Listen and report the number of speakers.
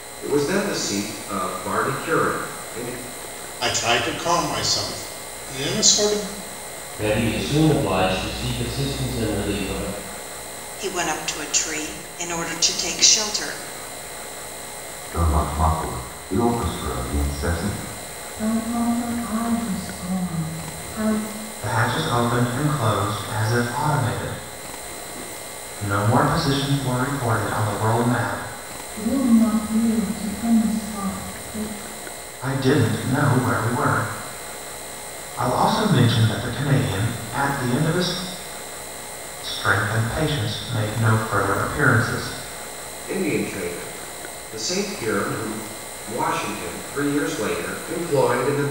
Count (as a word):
seven